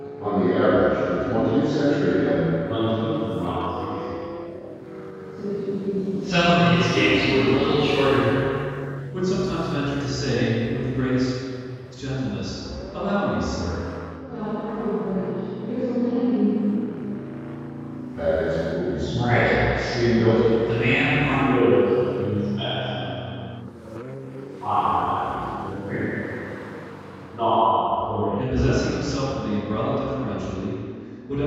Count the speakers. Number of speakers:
five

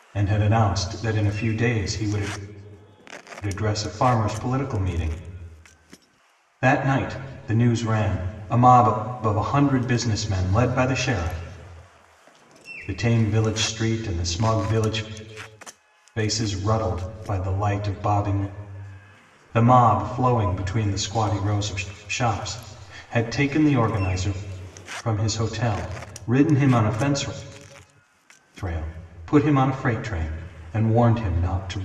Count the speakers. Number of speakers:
one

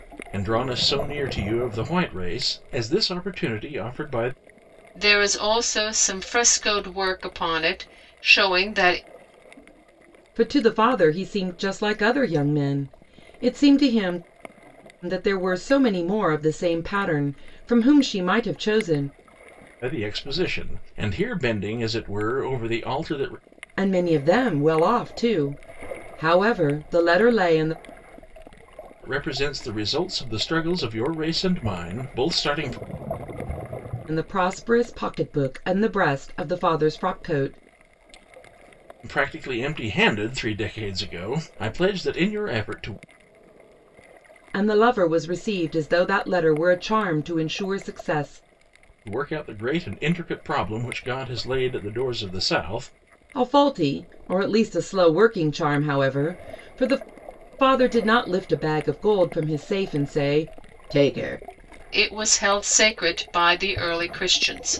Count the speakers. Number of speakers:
three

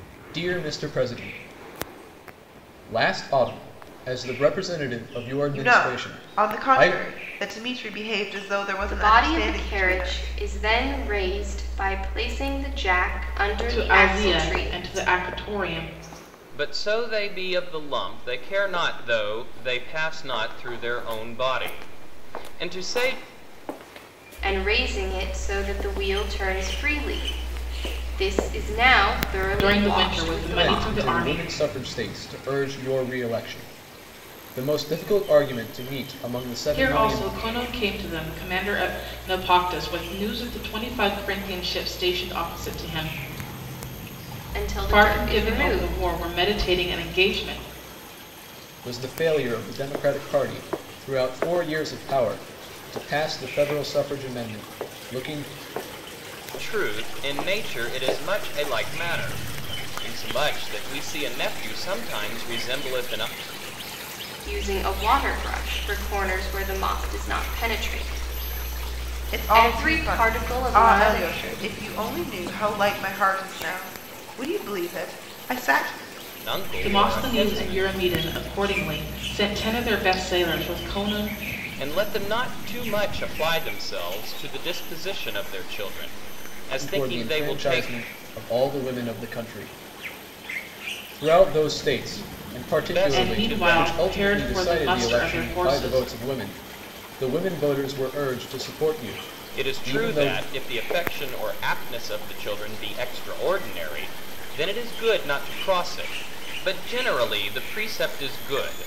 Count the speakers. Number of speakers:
five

